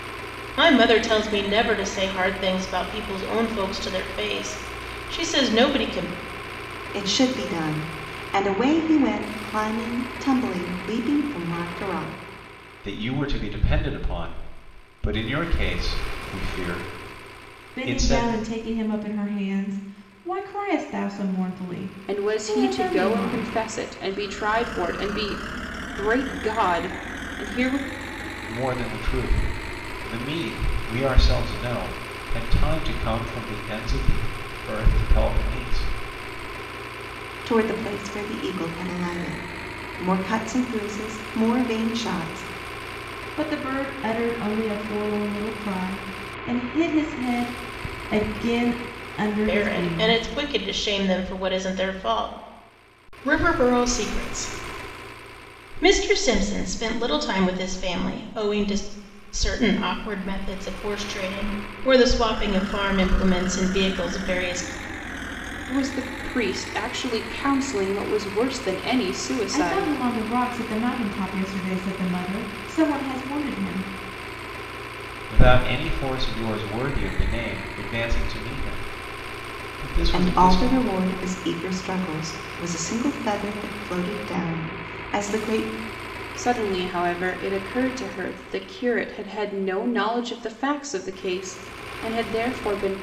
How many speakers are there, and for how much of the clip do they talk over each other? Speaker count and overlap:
five, about 5%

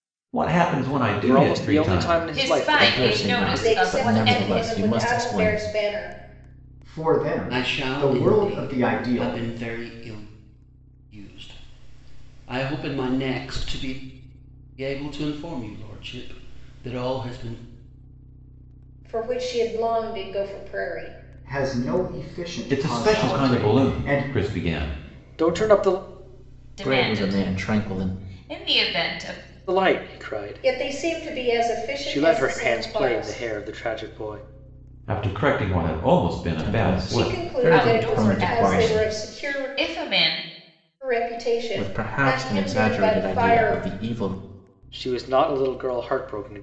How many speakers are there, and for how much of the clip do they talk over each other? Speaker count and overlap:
seven, about 40%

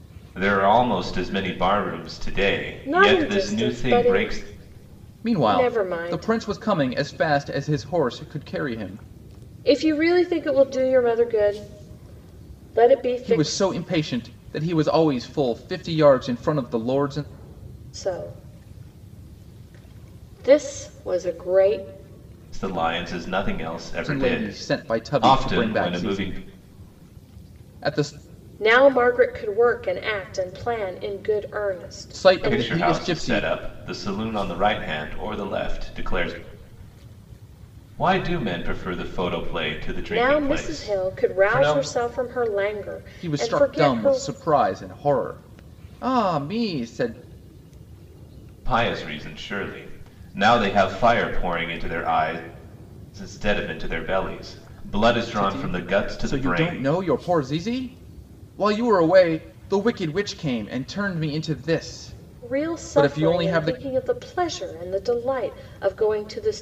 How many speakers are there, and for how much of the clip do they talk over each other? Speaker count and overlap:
three, about 19%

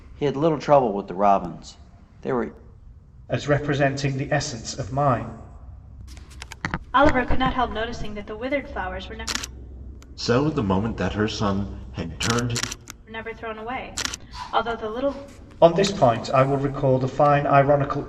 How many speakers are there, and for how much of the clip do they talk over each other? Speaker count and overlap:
four, no overlap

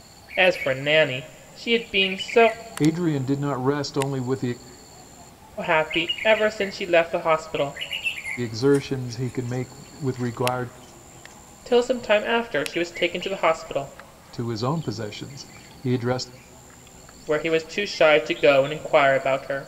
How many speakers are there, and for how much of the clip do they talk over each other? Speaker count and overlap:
two, no overlap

